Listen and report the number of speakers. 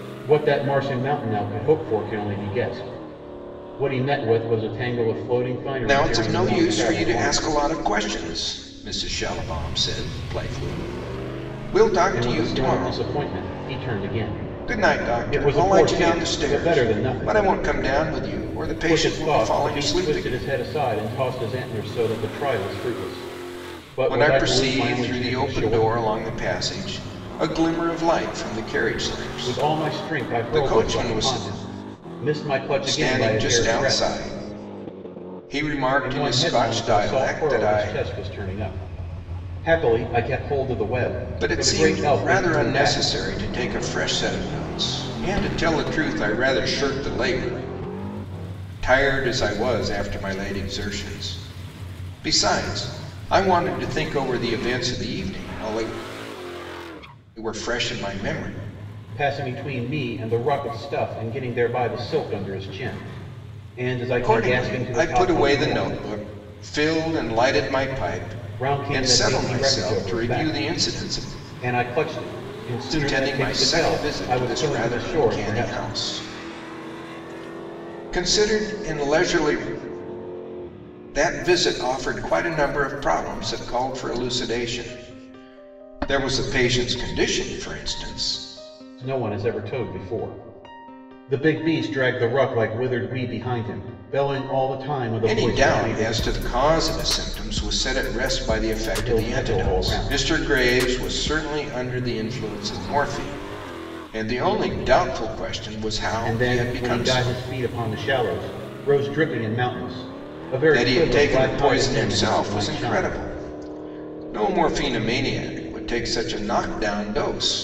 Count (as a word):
two